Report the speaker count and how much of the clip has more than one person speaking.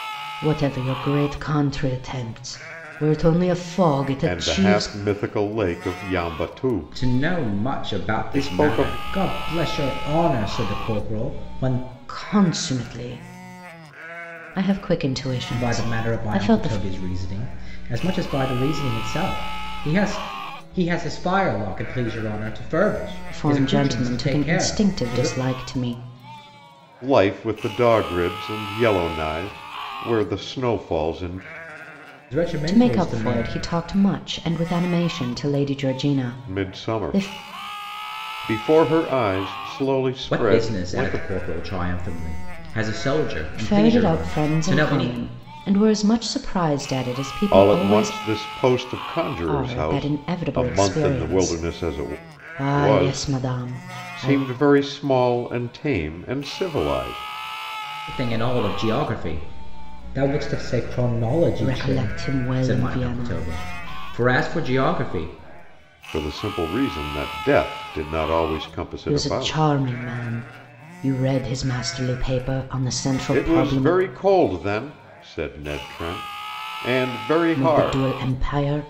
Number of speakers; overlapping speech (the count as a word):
three, about 25%